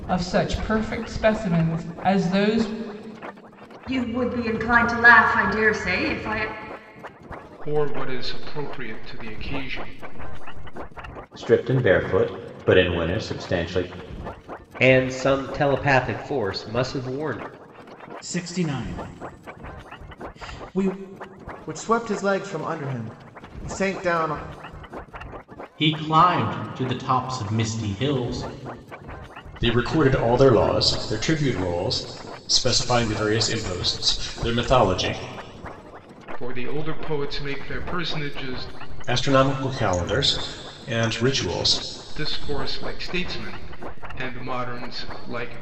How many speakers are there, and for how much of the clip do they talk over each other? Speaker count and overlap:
9, no overlap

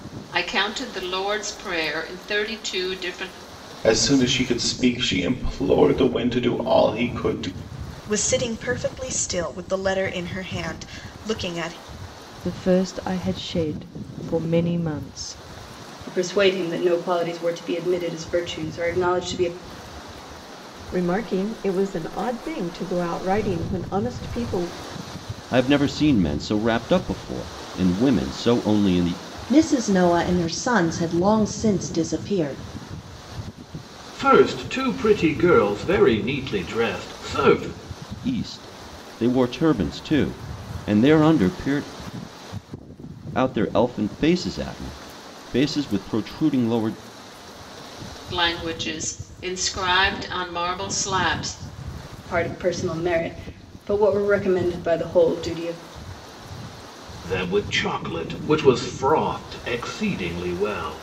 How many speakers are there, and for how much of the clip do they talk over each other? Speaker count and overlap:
9, no overlap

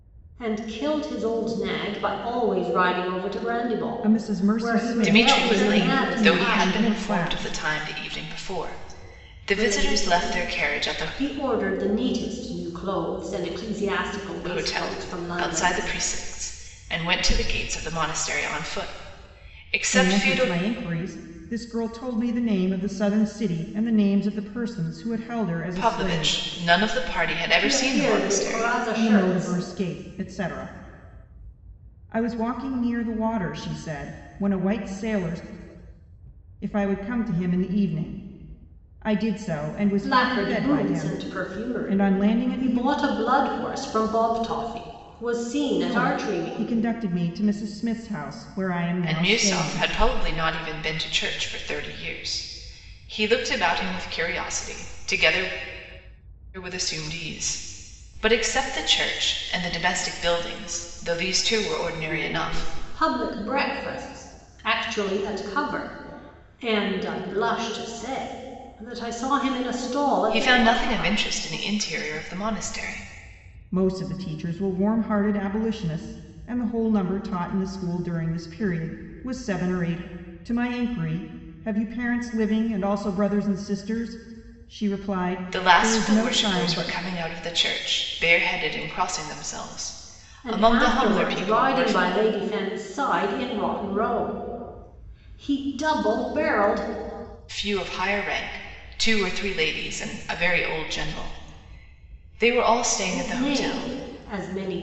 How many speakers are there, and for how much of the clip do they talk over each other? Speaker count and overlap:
3, about 19%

